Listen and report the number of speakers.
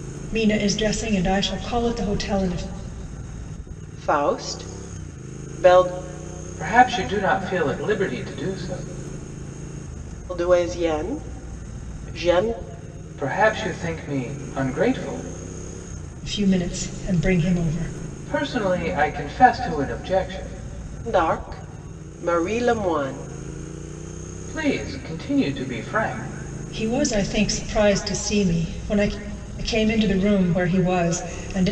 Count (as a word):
three